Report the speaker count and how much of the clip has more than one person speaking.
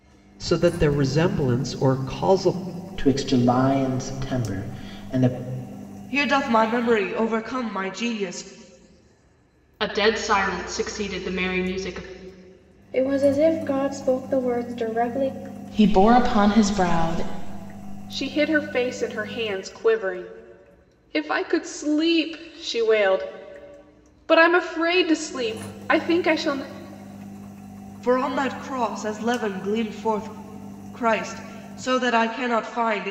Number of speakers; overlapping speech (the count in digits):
7, no overlap